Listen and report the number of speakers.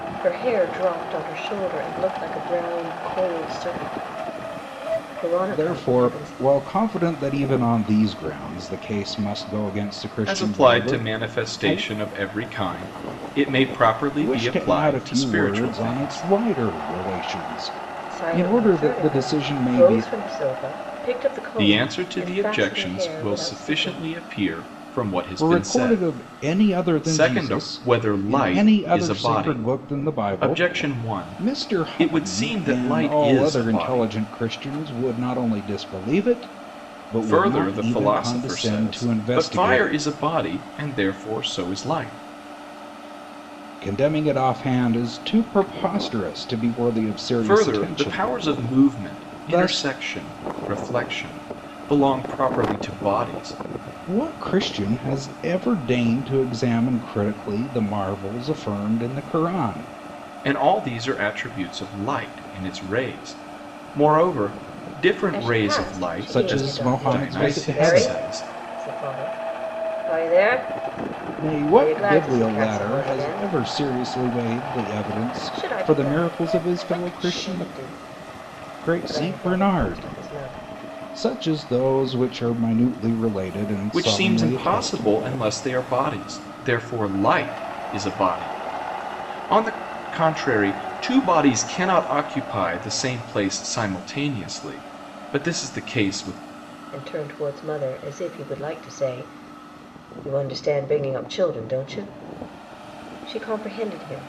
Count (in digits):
3